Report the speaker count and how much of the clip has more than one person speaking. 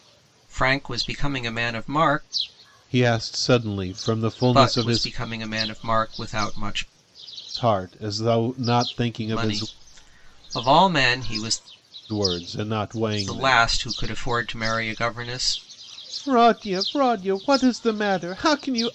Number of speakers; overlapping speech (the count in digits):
2, about 8%